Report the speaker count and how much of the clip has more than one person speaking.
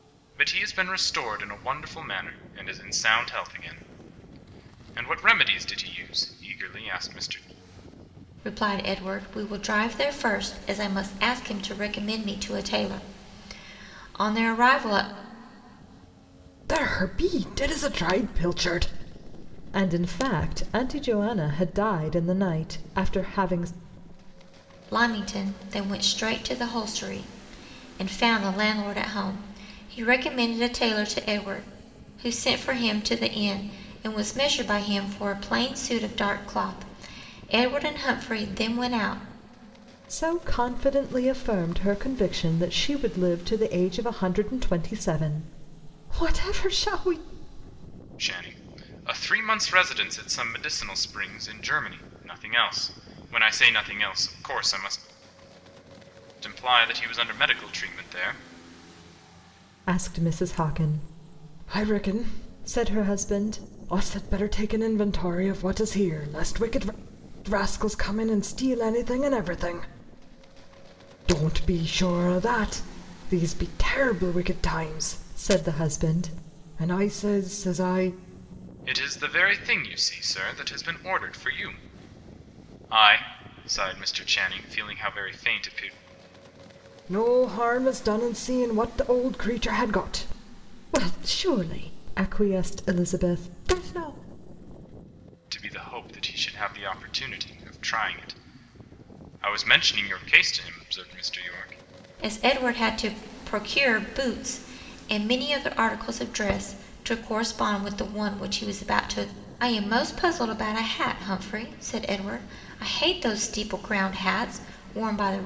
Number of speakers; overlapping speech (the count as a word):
three, no overlap